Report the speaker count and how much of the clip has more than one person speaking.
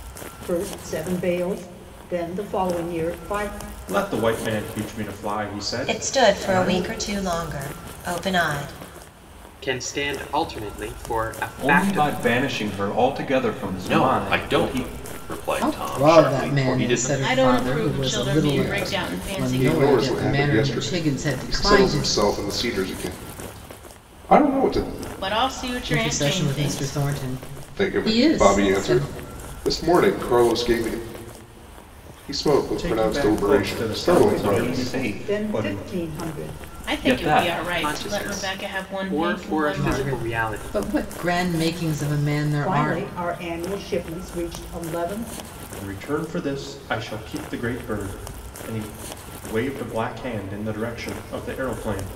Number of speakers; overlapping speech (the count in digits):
9, about 38%